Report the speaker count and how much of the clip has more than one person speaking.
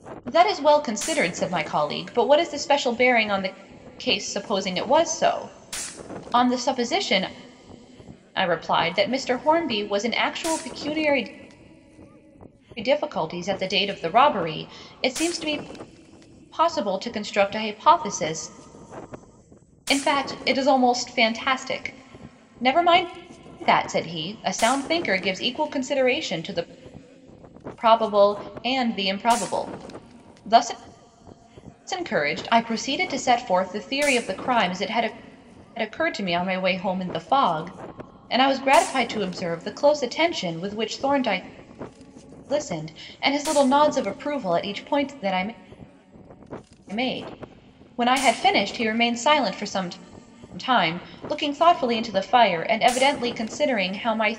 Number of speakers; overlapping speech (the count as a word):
one, no overlap